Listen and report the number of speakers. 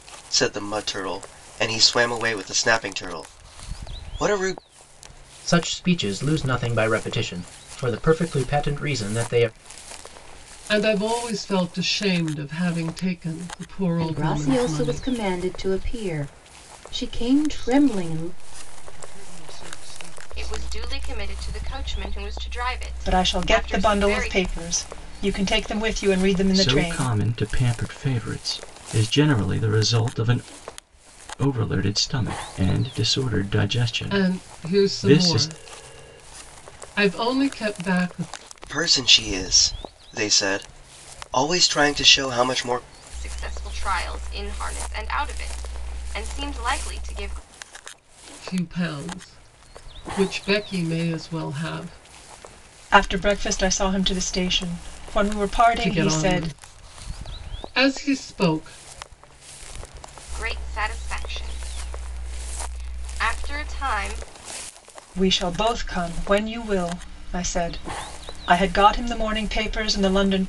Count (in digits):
8